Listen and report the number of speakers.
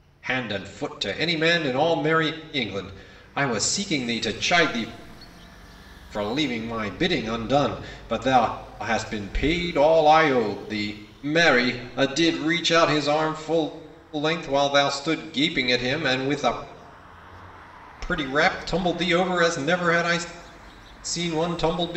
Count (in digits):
1